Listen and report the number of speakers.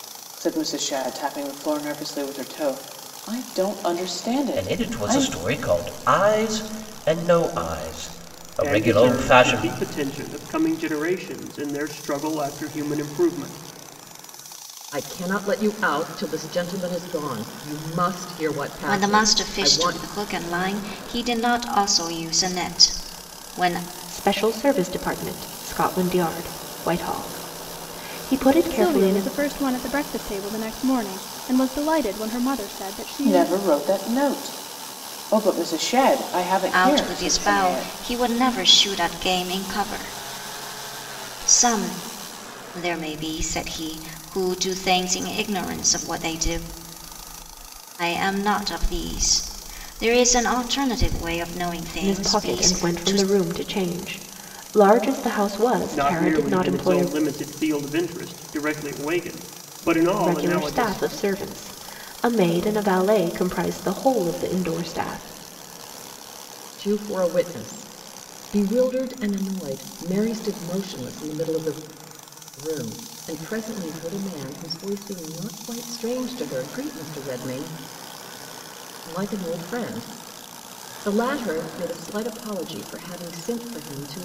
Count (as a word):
seven